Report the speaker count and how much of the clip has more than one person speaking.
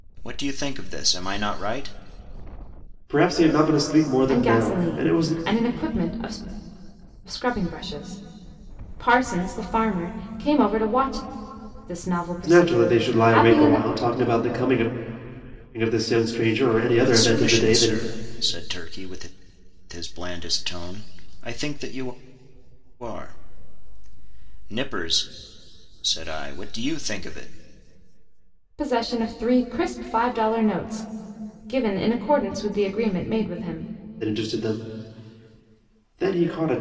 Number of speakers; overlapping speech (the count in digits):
3, about 10%